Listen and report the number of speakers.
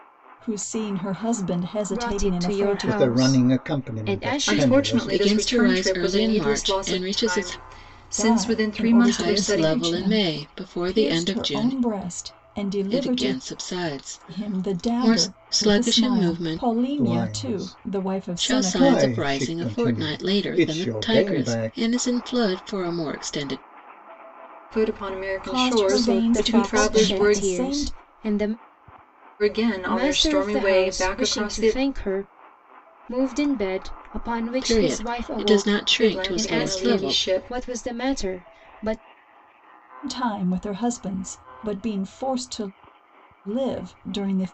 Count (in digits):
5